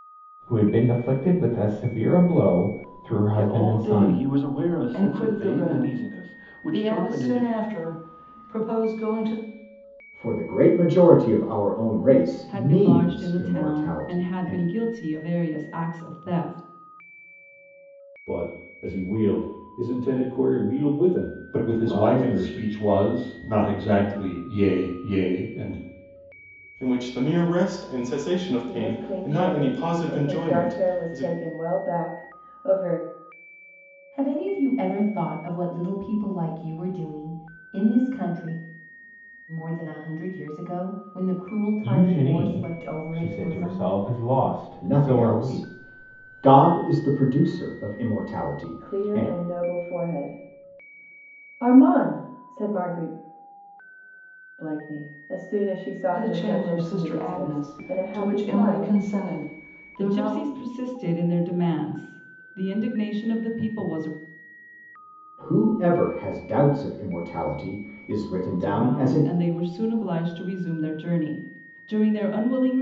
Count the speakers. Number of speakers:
ten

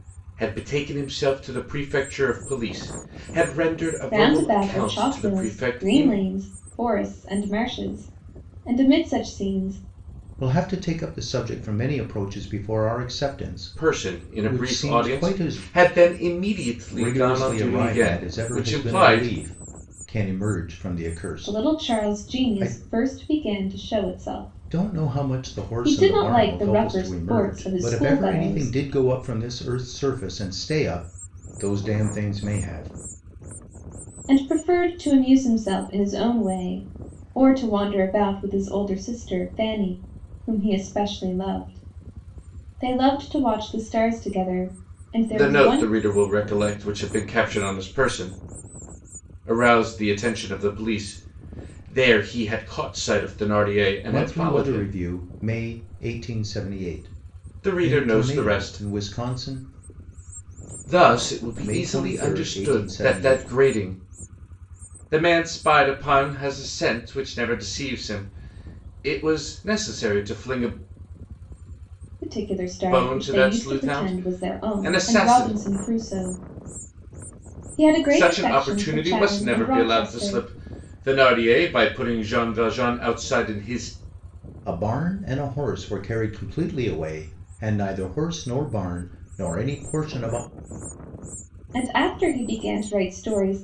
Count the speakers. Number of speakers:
three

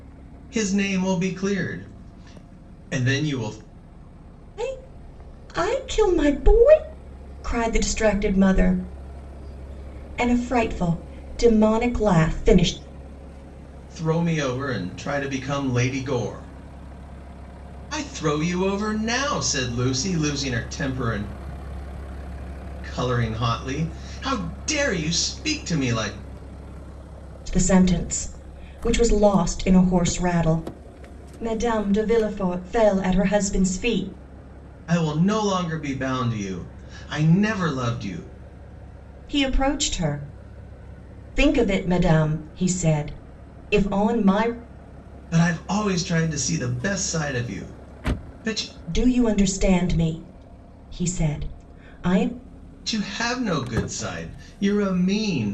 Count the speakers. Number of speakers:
two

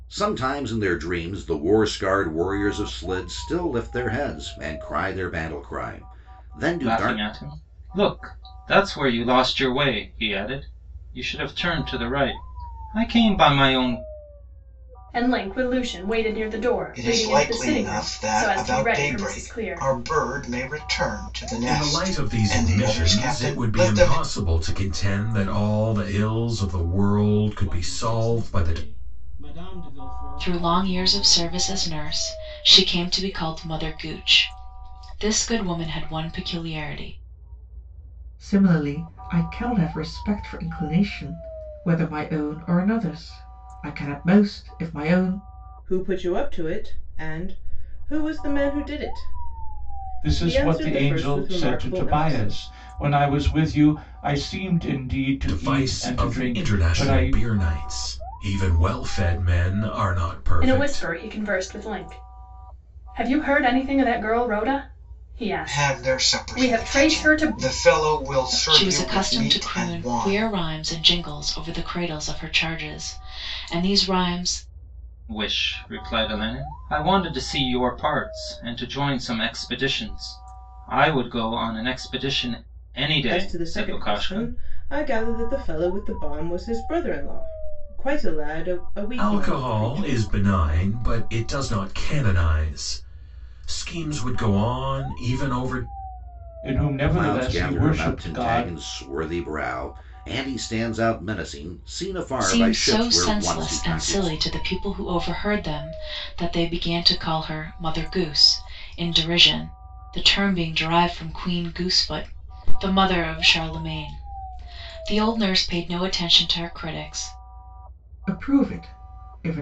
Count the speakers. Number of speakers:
ten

